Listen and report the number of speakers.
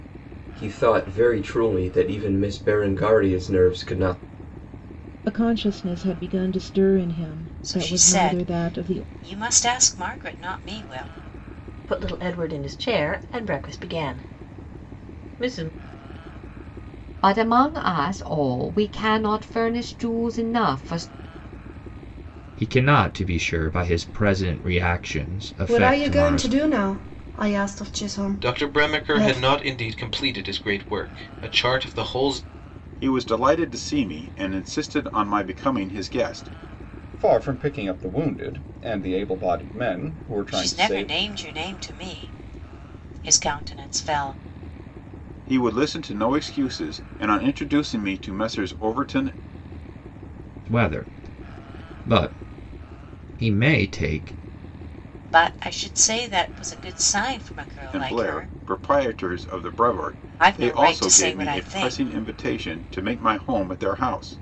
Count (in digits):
10